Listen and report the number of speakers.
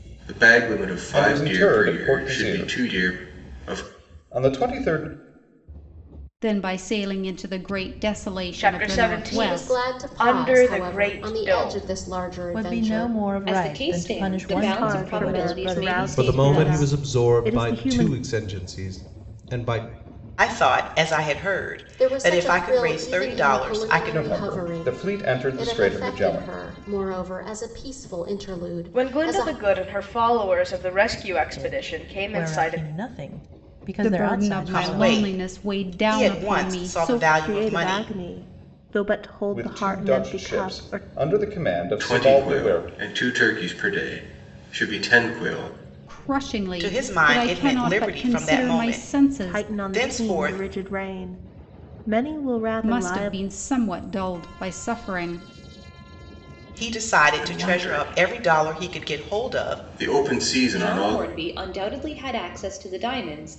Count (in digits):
10